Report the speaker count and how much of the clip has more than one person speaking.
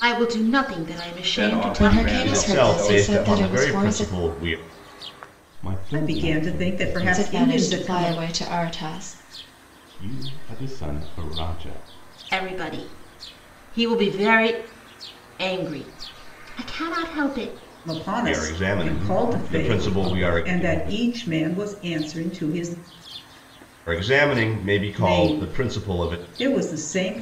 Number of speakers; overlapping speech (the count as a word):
six, about 33%